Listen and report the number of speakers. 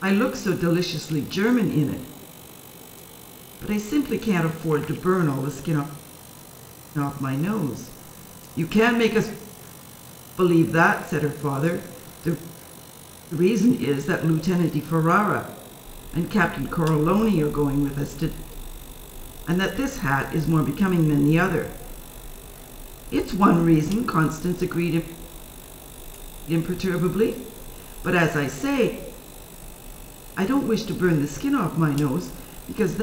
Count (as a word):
one